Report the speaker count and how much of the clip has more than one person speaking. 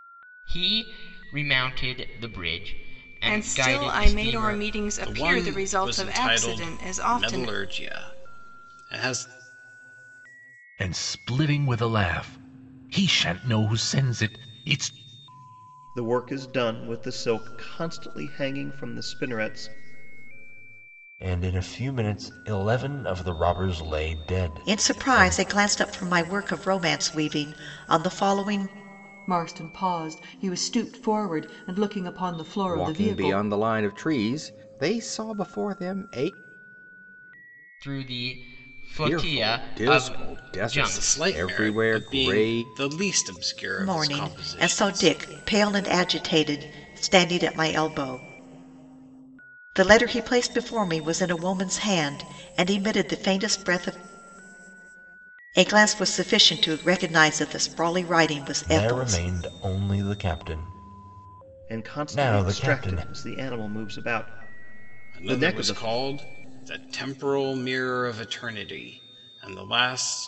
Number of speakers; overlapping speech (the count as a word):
nine, about 19%